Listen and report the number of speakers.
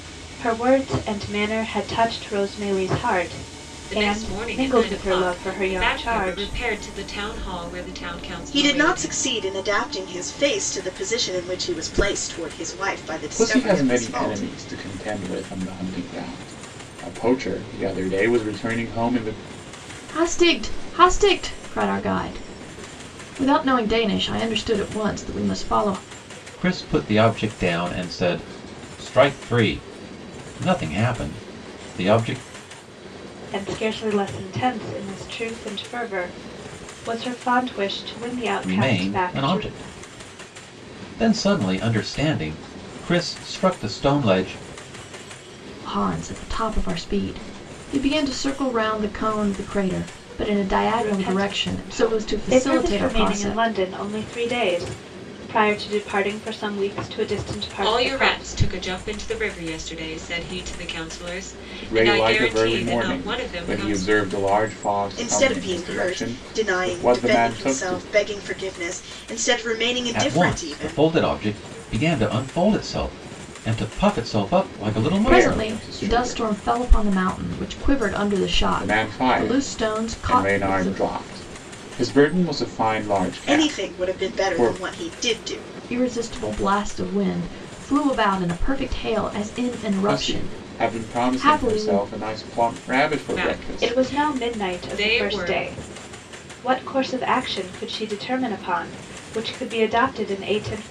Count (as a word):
six